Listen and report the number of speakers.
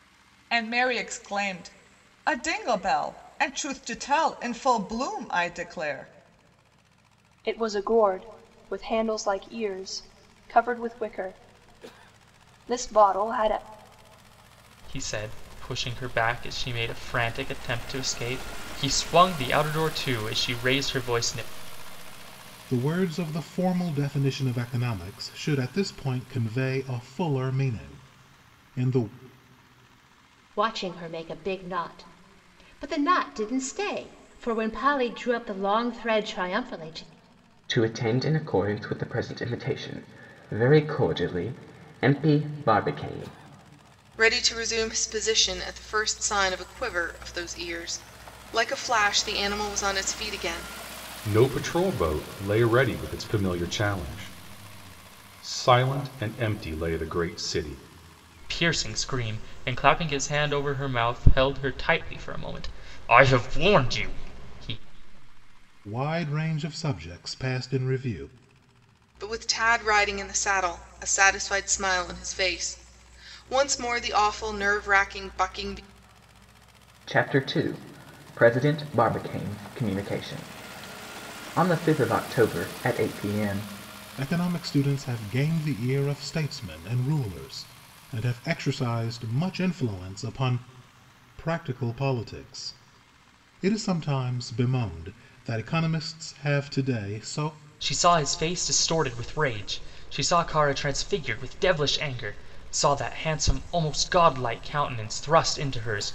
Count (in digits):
8